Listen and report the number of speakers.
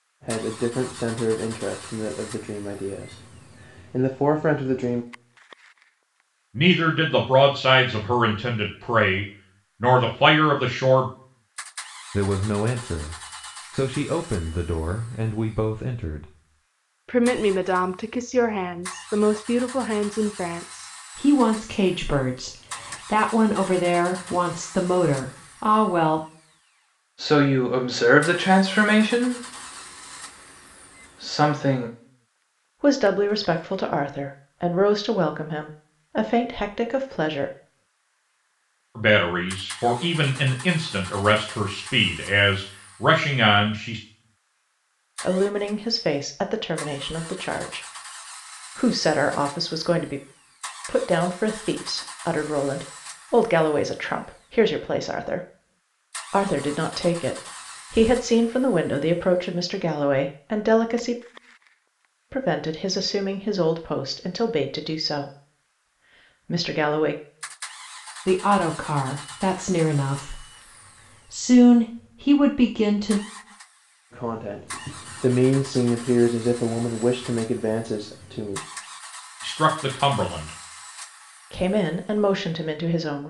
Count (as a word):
seven